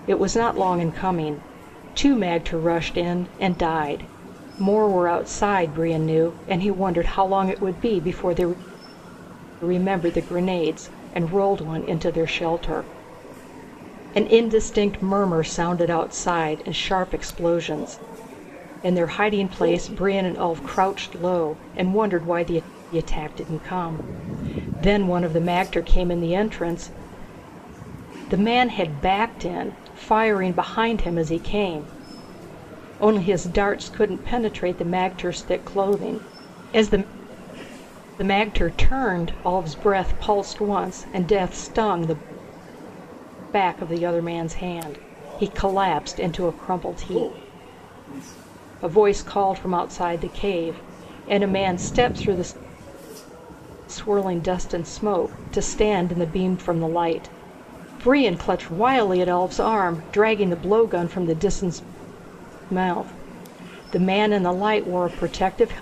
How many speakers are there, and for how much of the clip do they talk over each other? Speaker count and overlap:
one, no overlap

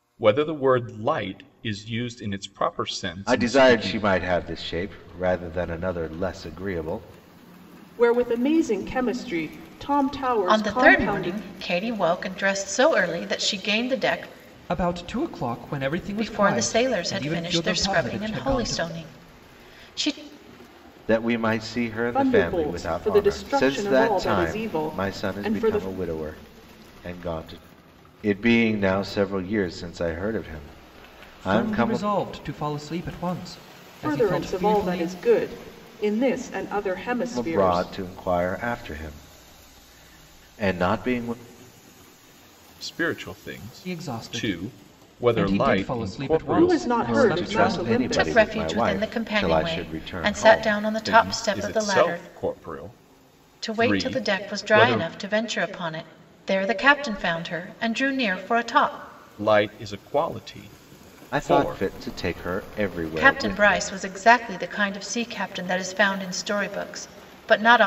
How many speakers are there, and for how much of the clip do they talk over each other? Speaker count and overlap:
five, about 32%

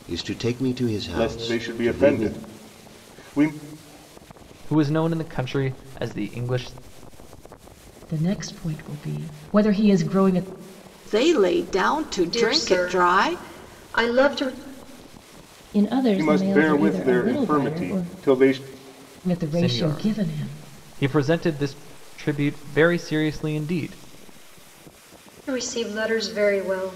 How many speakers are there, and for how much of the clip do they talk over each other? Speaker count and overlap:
seven, about 20%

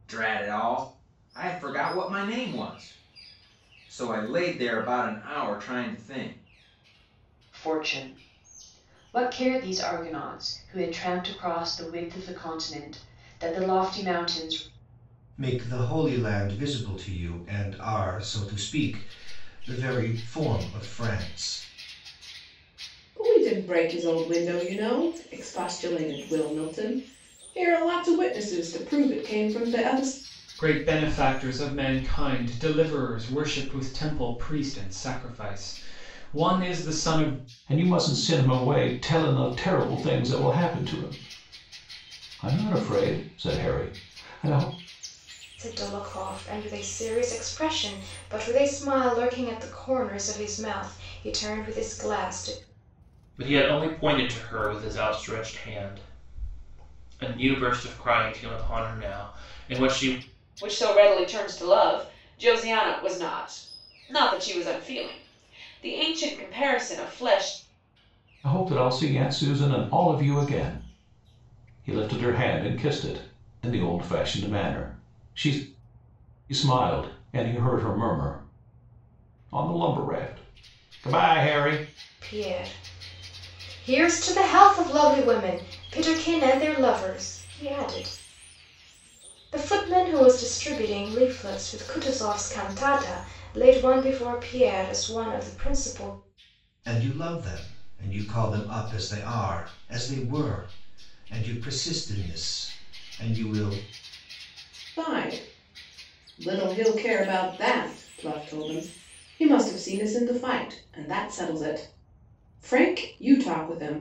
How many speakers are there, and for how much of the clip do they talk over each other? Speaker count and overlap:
nine, no overlap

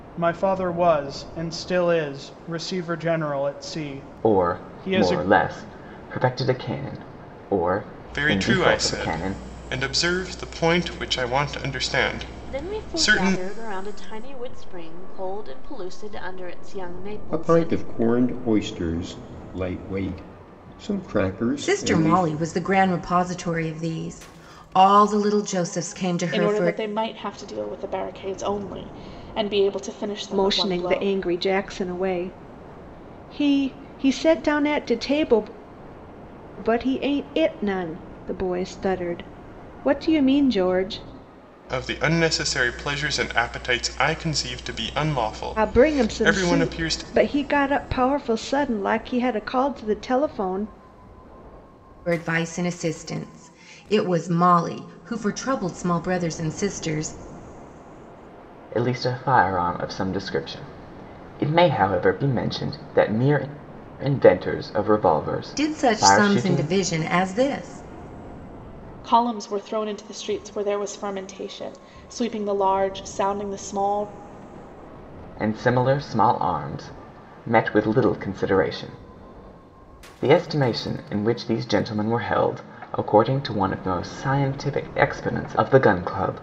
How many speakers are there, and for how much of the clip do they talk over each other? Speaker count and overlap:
eight, about 10%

